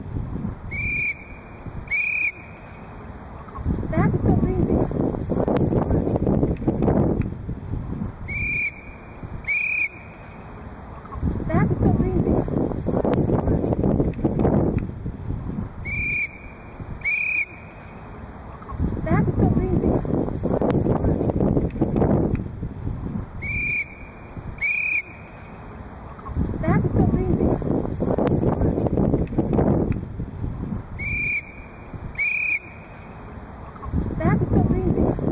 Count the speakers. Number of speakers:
zero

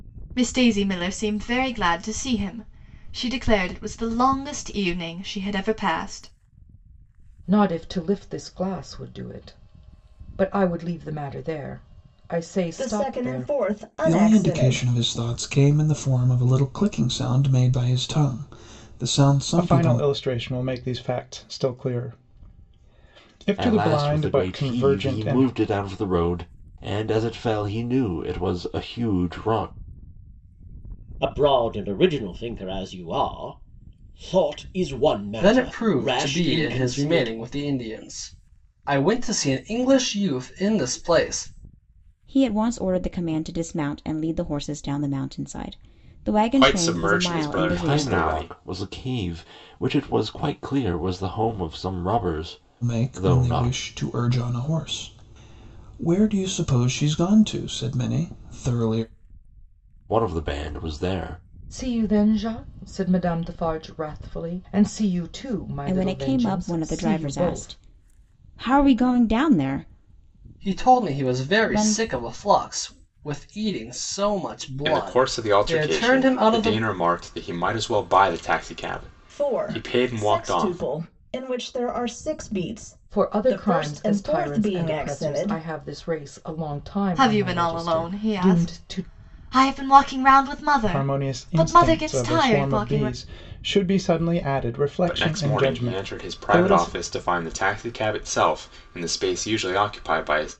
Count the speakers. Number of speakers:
ten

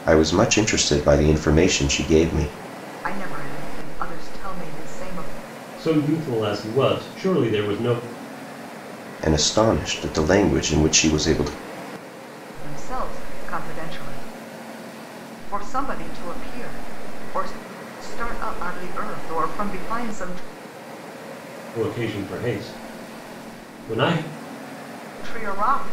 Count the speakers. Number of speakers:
three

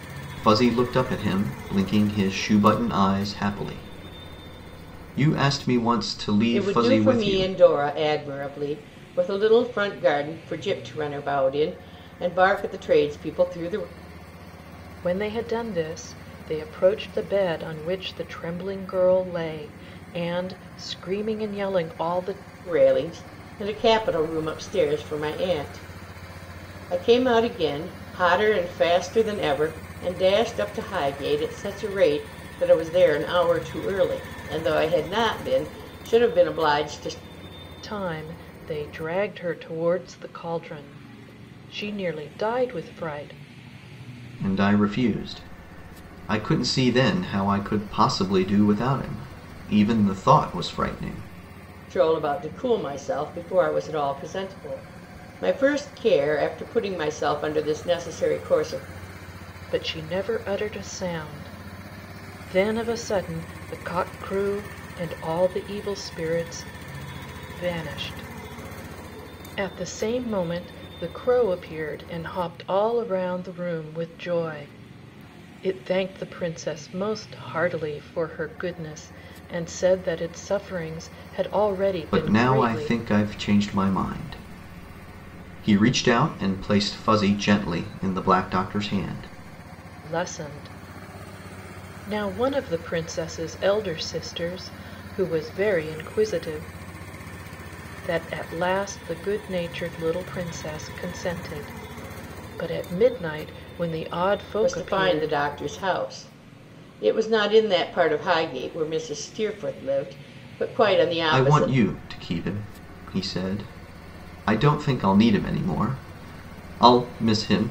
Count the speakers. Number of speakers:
three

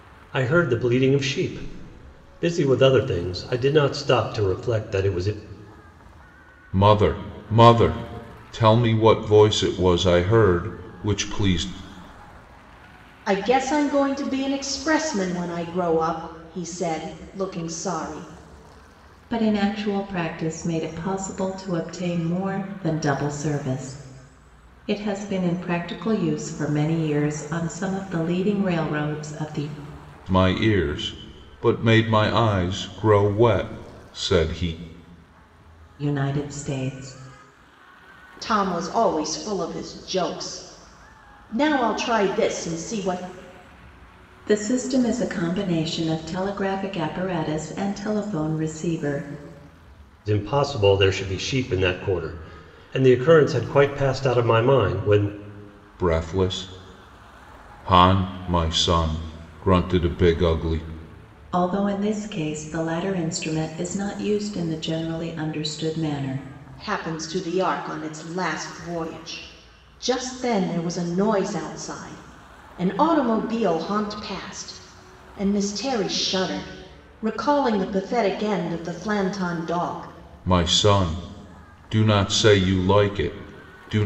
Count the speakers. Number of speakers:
four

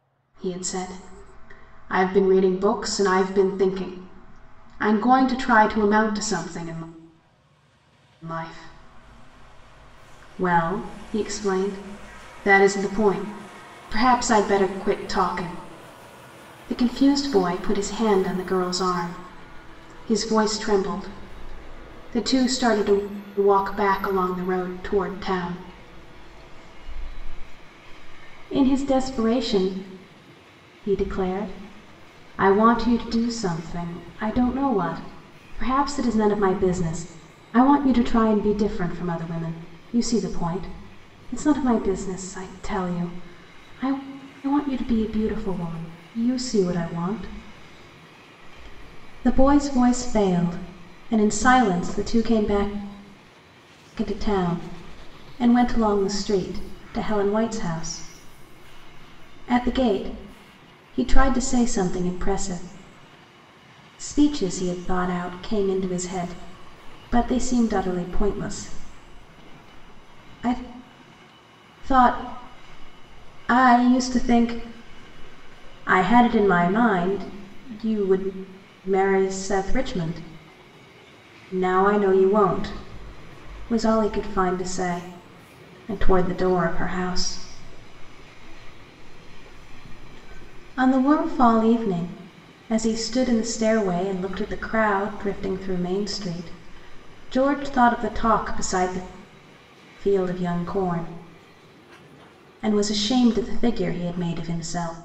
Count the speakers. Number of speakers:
one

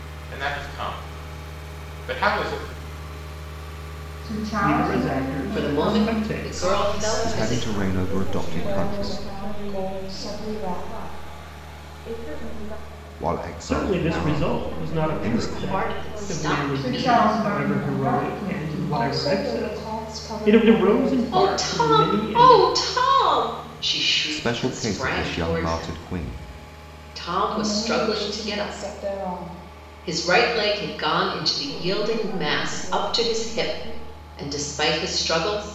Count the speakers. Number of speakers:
eight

